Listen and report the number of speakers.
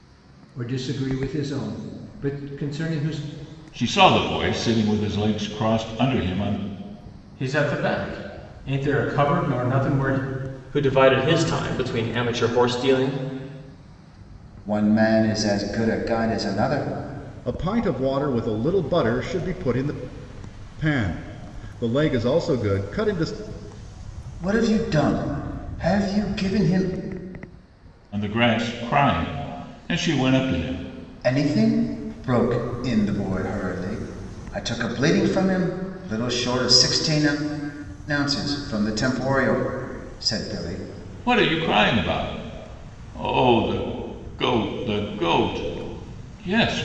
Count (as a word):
six